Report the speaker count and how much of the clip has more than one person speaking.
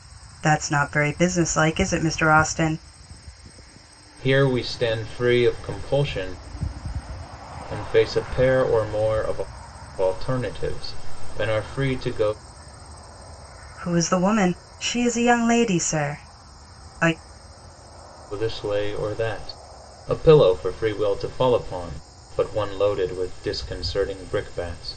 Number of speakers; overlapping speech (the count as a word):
two, no overlap